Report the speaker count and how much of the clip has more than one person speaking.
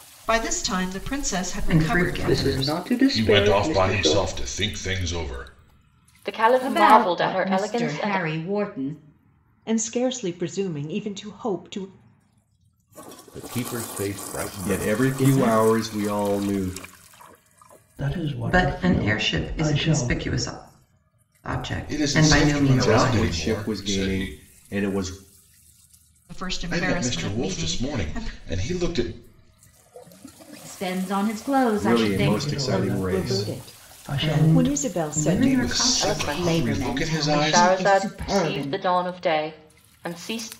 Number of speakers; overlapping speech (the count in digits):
10, about 44%